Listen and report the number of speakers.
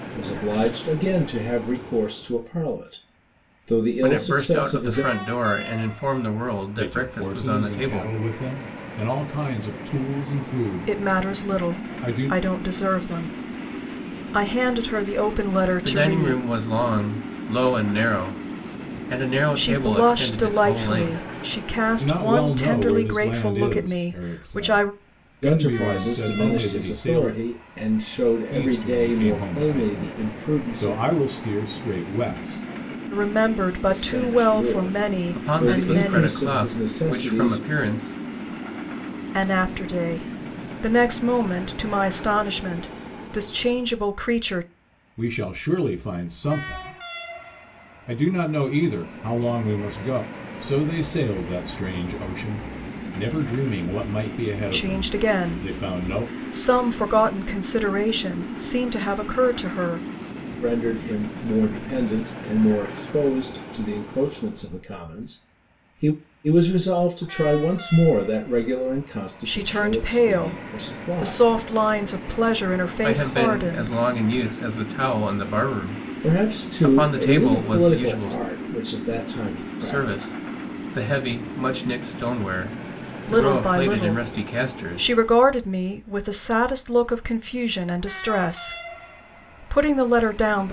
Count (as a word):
four